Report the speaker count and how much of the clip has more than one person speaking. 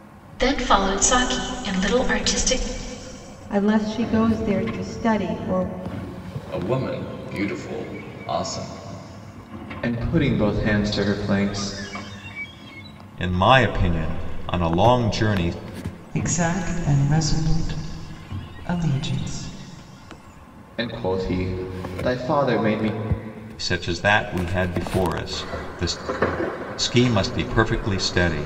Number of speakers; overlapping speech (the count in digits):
6, no overlap